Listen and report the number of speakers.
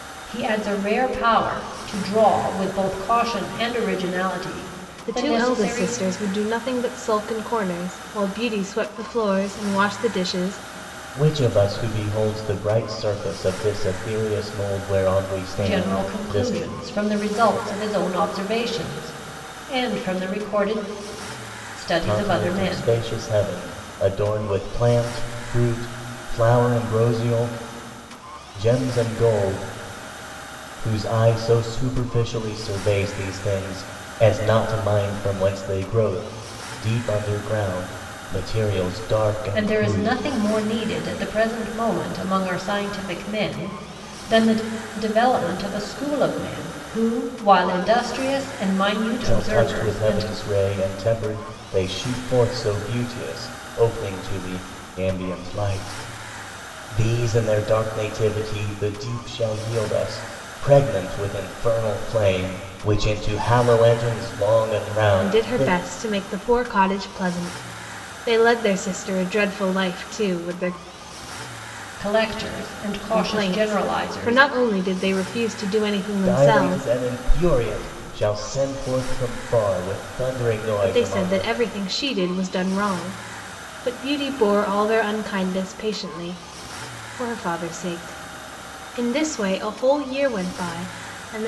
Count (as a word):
three